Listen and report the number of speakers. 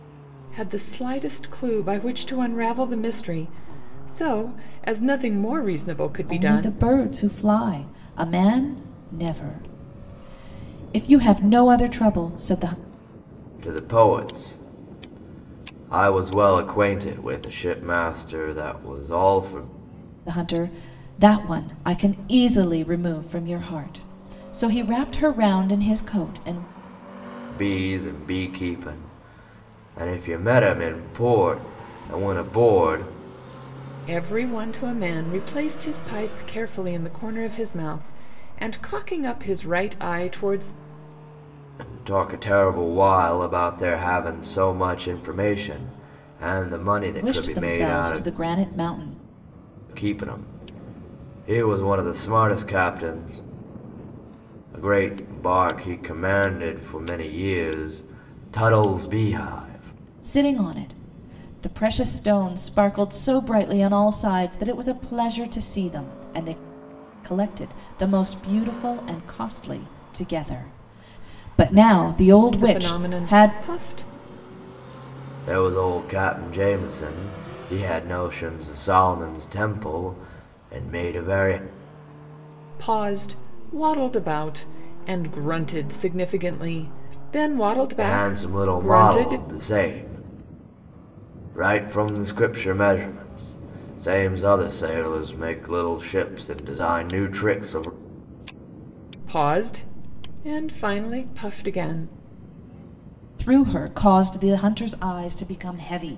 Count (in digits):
3